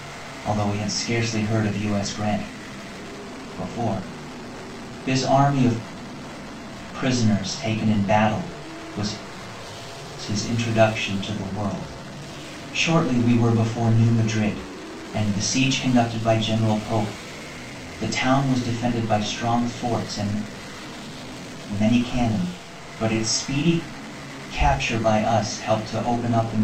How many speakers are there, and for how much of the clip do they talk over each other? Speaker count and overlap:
1, no overlap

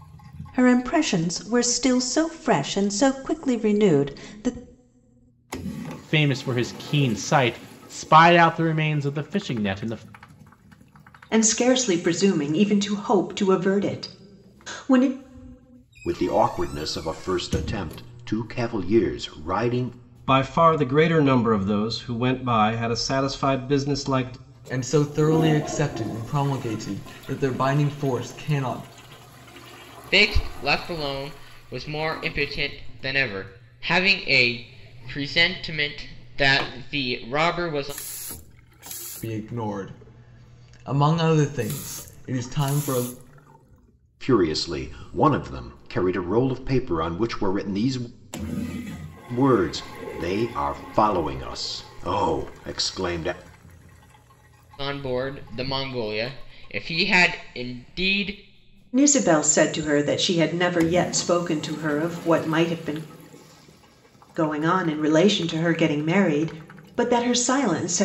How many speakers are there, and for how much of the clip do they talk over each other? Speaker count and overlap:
7, no overlap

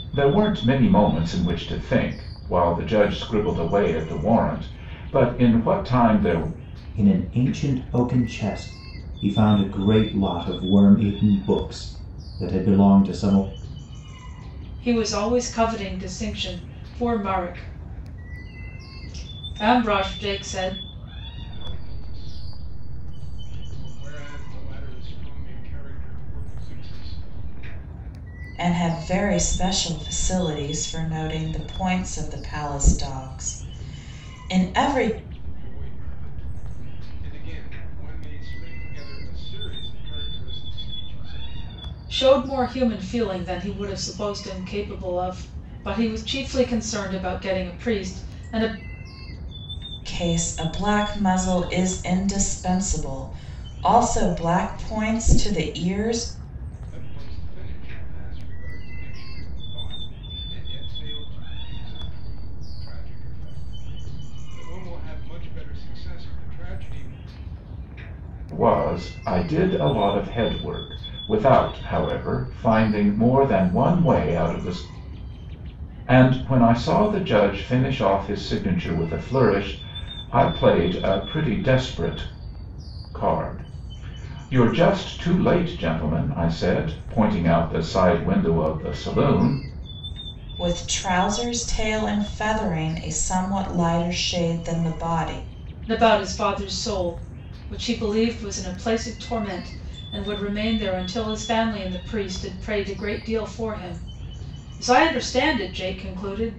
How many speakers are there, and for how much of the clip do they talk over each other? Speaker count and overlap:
5, no overlap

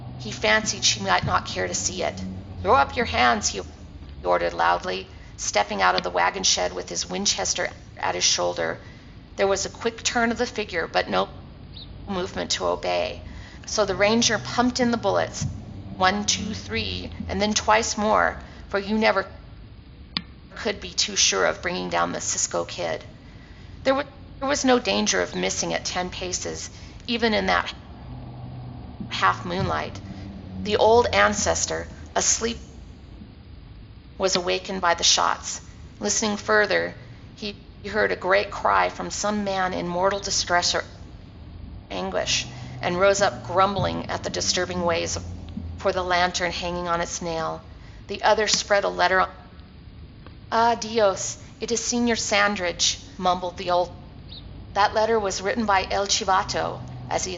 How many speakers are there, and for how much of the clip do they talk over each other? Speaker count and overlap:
1, no overlap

